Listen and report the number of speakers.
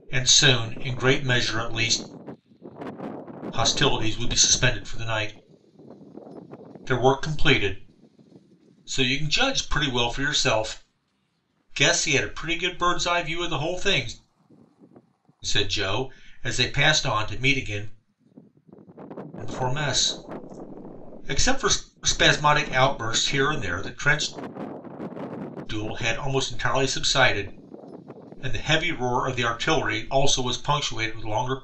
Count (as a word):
one